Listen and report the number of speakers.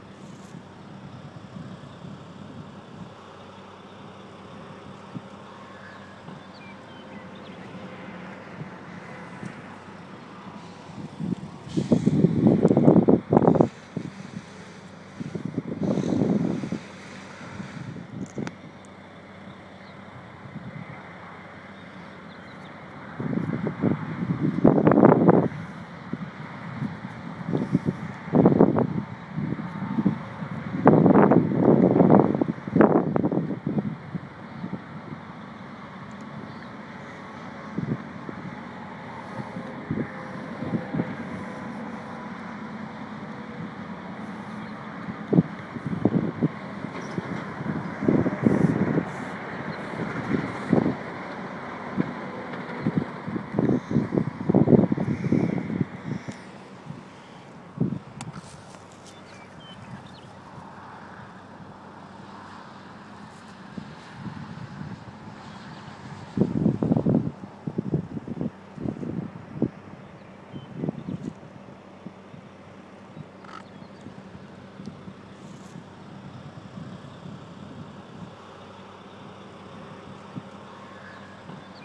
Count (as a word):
zero